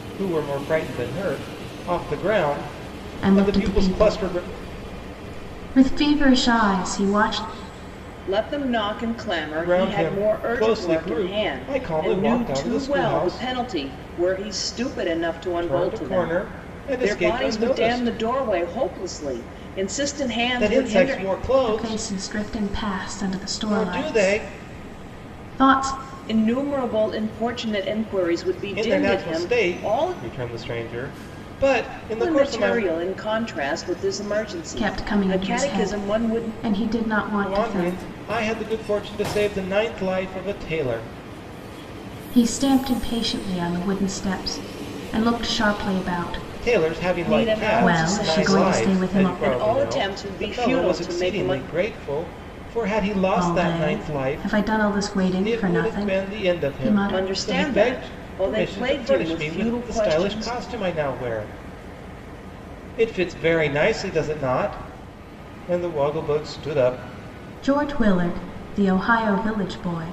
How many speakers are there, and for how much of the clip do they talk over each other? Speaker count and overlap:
3, about 38%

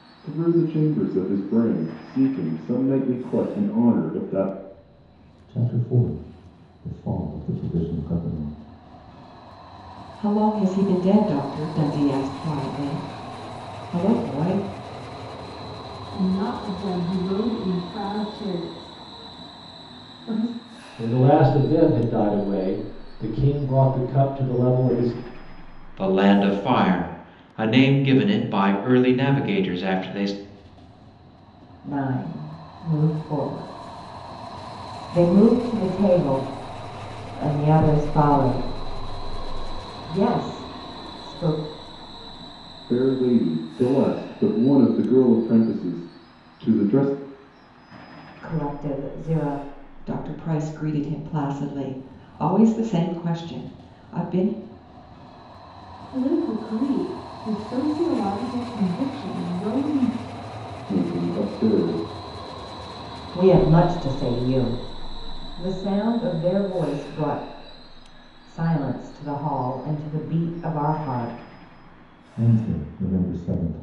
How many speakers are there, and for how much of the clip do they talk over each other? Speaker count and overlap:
7, no overlap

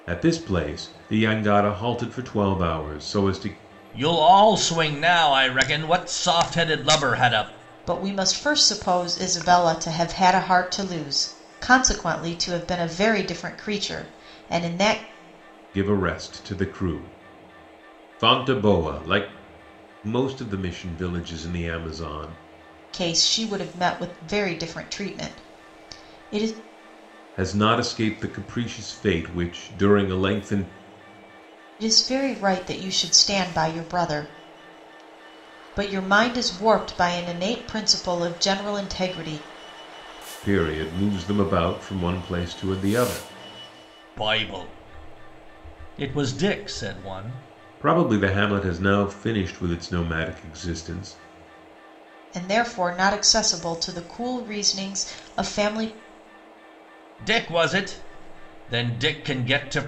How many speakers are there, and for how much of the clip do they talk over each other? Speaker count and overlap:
3, no overlap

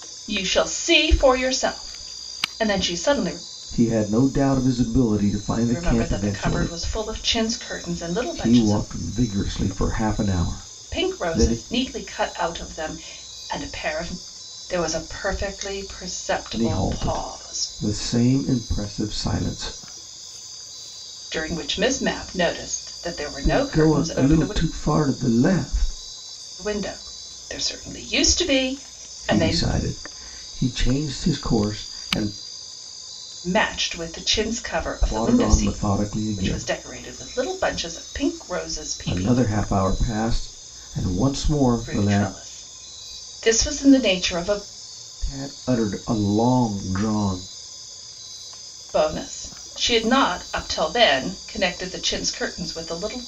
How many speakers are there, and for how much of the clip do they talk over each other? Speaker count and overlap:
2, about 14%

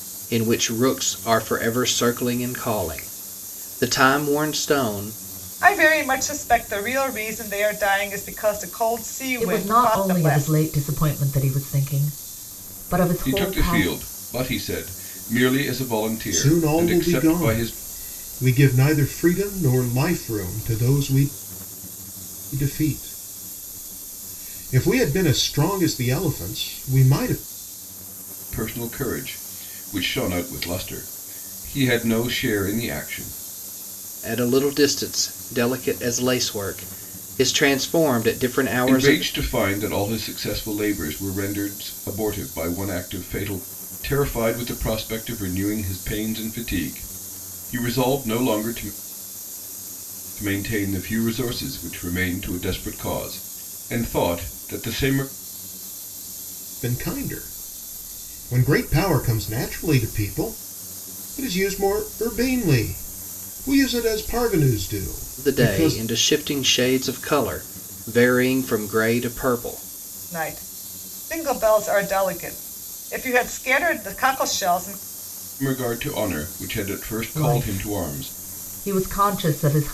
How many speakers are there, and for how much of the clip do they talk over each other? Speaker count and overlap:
5, about 7%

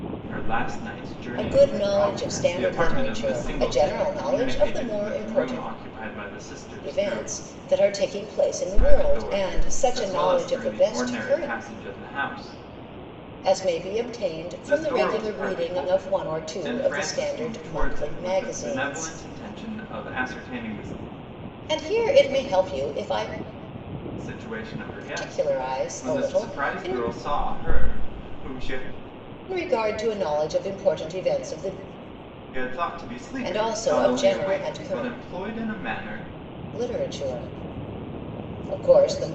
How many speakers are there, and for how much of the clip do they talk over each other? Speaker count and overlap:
2, about 40%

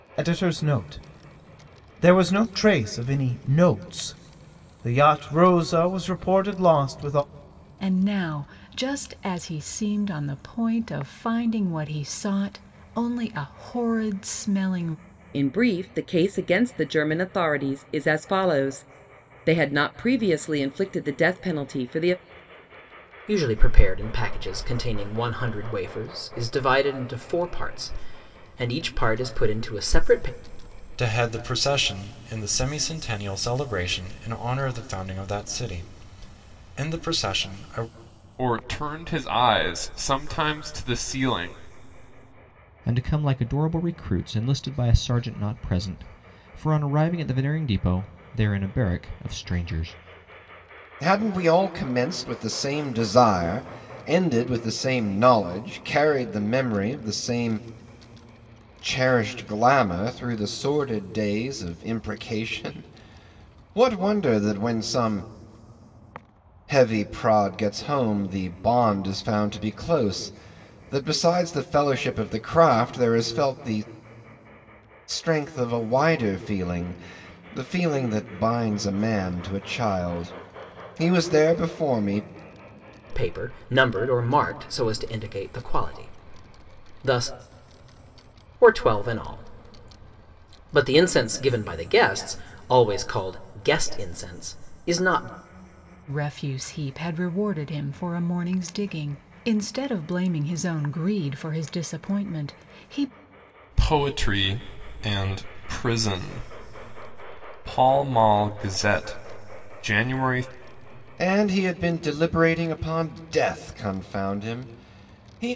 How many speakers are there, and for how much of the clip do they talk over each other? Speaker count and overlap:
8, no overlap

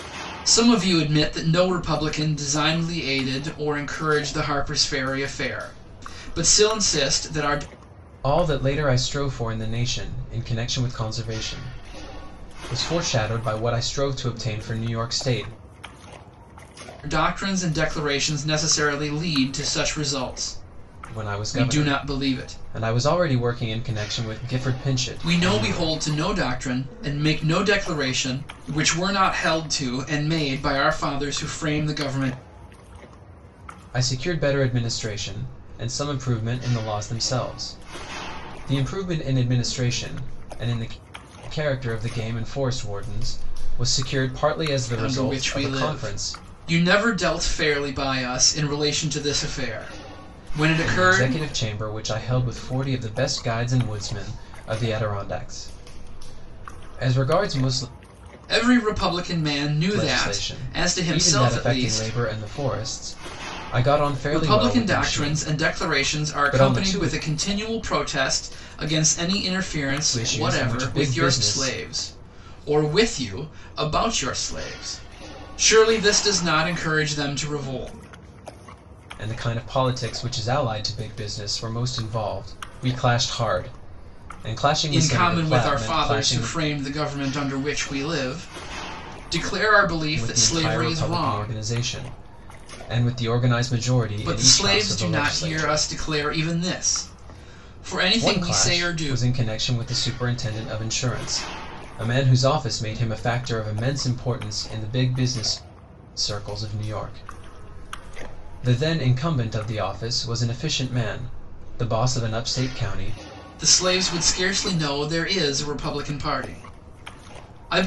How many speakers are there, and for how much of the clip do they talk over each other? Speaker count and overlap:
2, about 14%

